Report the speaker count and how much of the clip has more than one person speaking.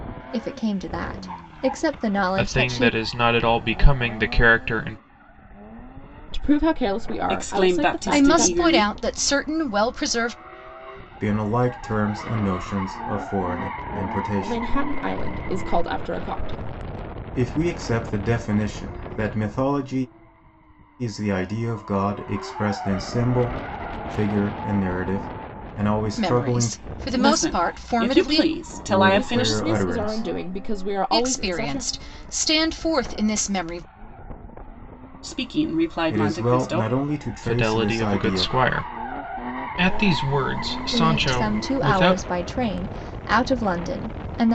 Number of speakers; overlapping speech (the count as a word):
six, about 22%